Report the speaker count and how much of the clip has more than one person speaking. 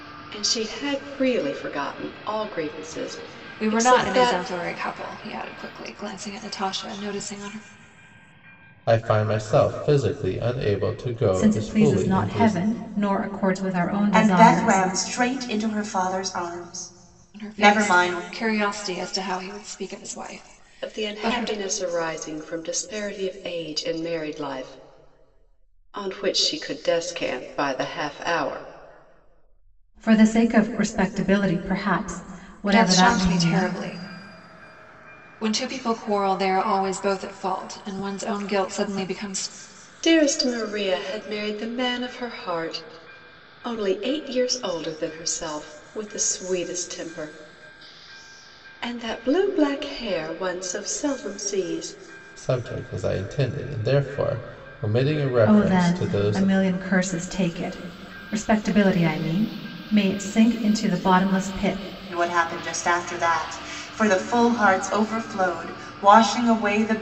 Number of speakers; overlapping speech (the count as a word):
five, about 10%